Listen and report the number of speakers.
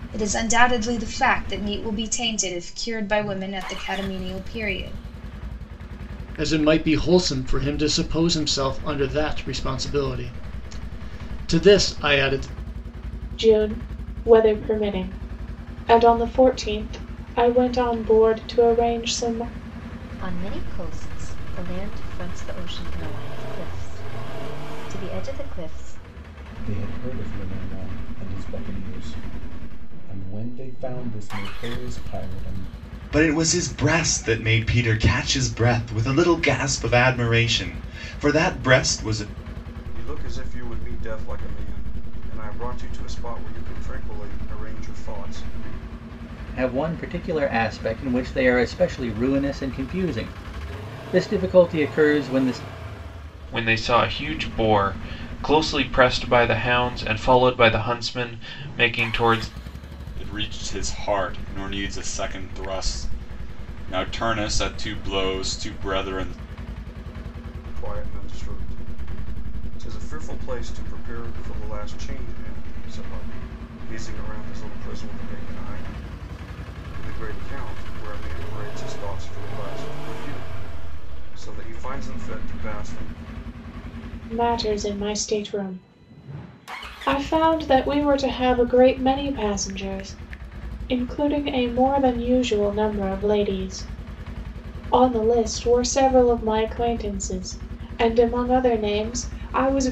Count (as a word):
ten